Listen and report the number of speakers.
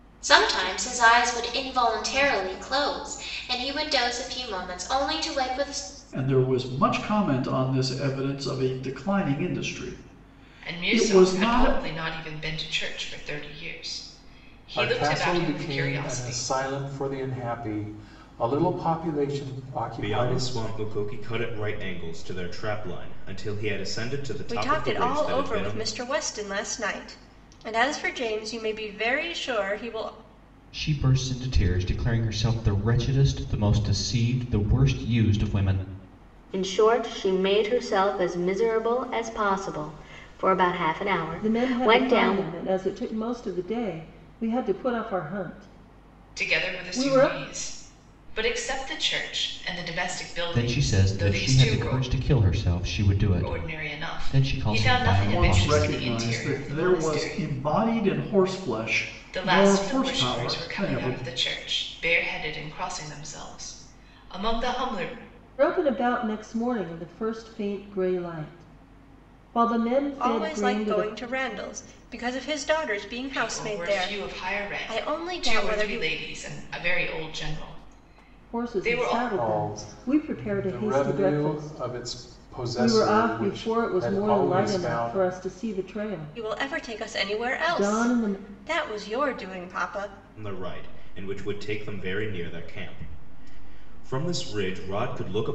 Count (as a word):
nine